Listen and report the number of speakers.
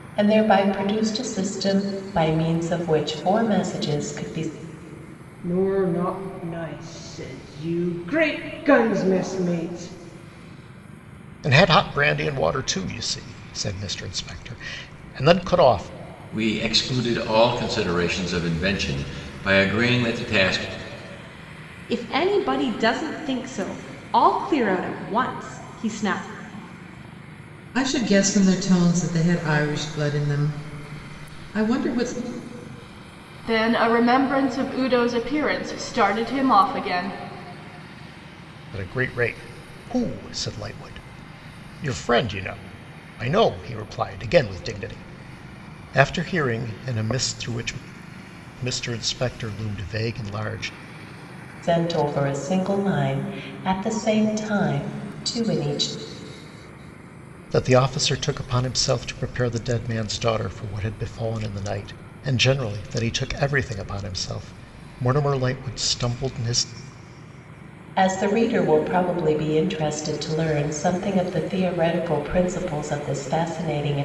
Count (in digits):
7